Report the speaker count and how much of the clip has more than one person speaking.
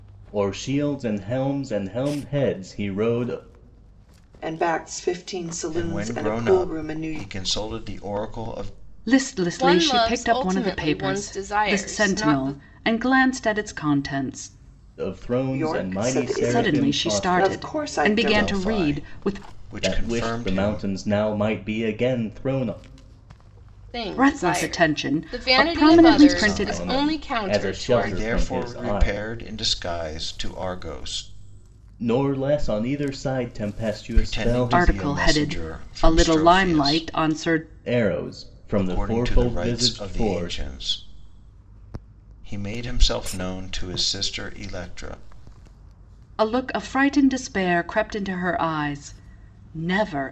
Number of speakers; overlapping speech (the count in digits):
5, about 38%